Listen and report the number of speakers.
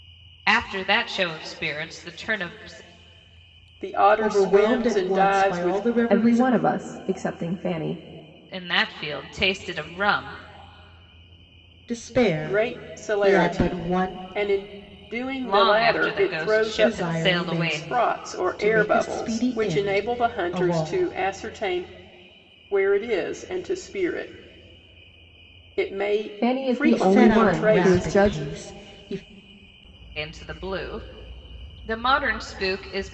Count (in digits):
4